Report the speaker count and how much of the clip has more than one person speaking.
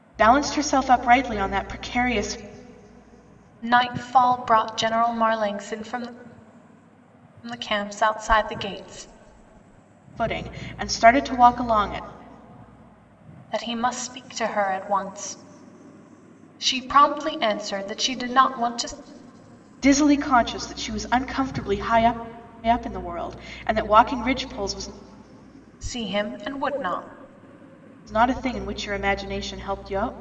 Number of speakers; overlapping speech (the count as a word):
two, no overlap